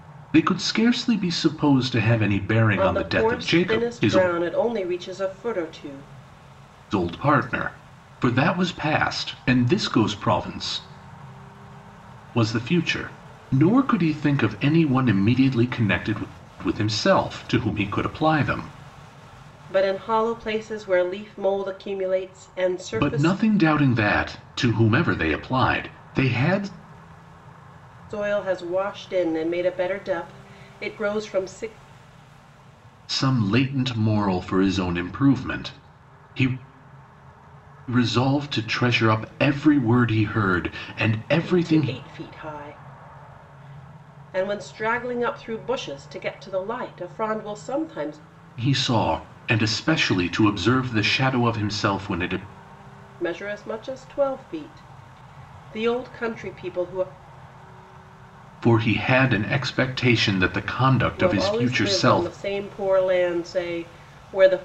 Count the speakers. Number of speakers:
two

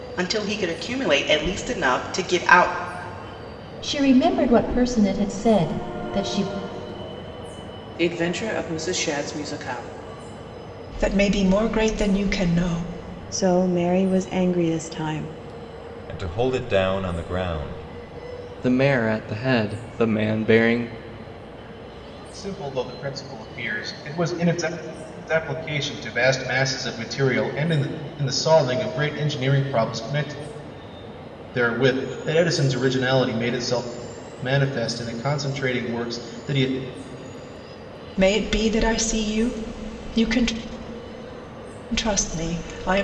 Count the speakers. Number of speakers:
eight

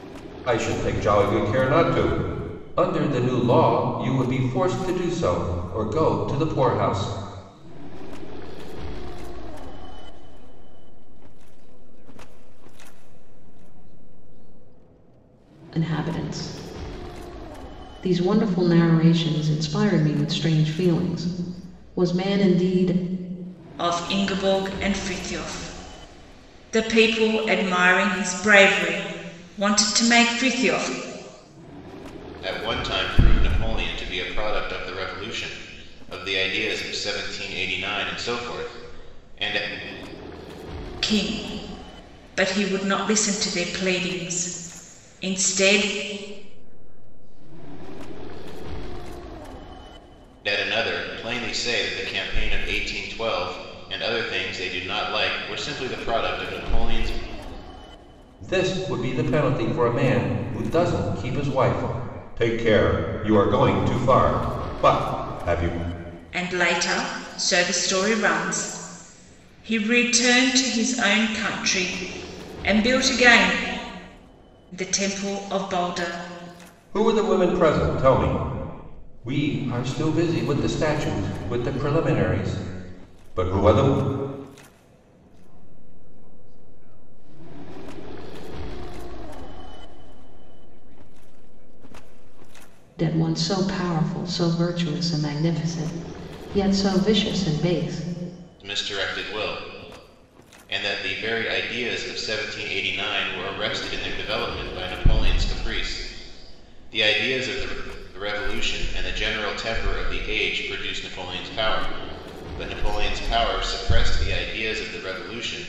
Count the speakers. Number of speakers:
five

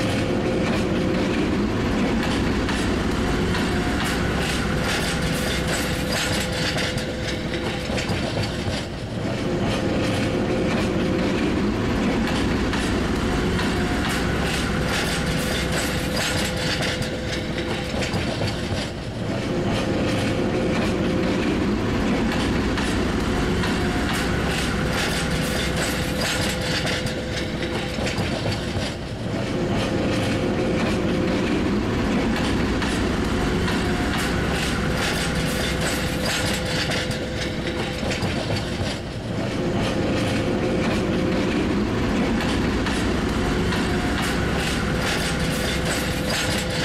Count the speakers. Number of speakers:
zero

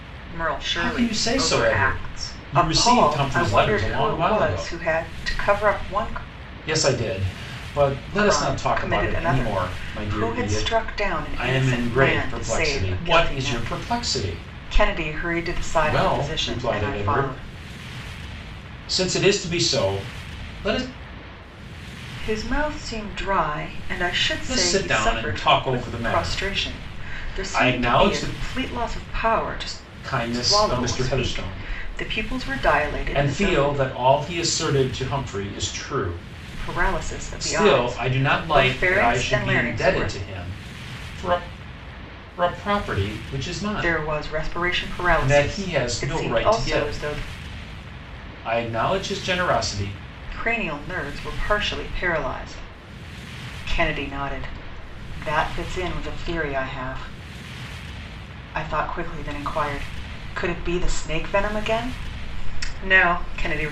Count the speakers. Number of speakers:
two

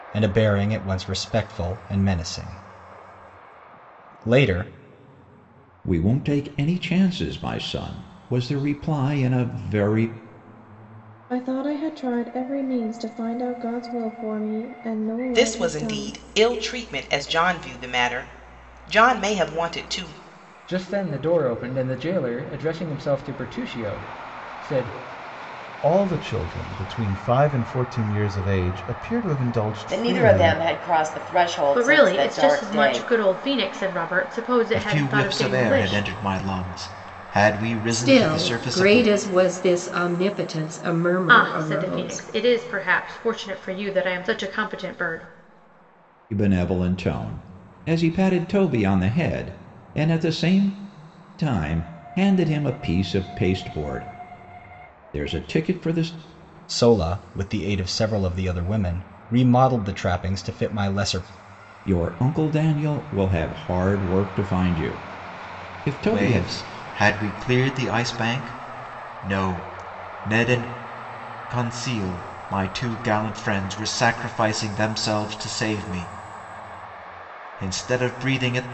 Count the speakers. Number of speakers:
ten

